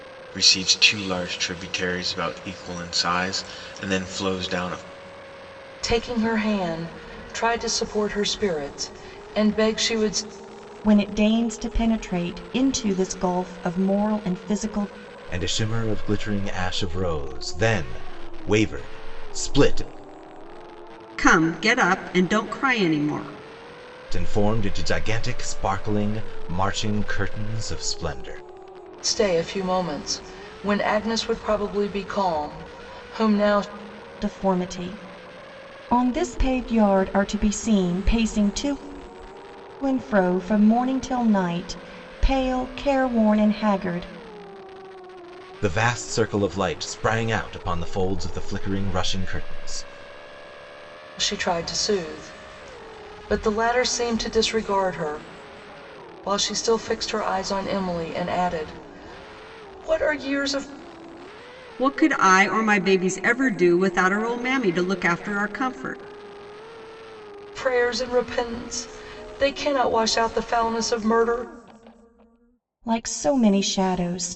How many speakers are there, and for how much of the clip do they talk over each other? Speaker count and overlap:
5, no overlap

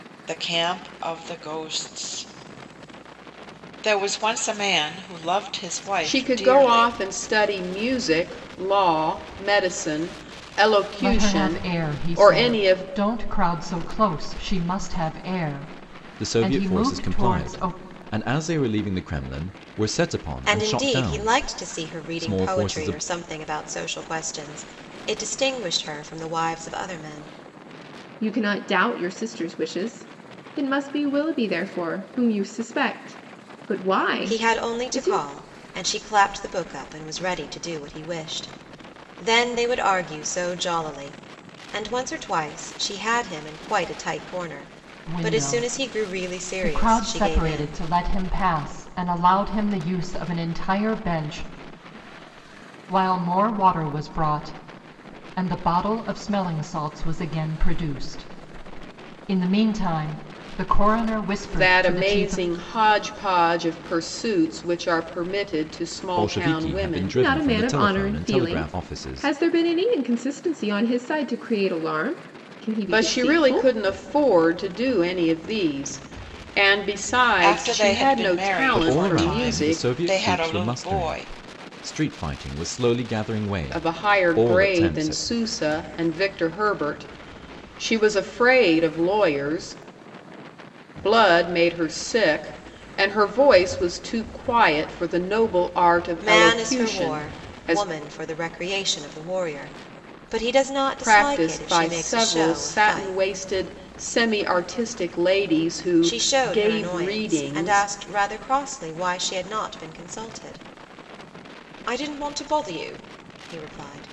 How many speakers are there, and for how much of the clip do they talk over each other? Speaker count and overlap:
6, about 24%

